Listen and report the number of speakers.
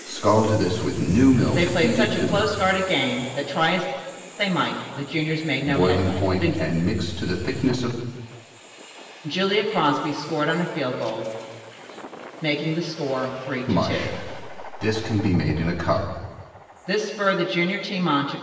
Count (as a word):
two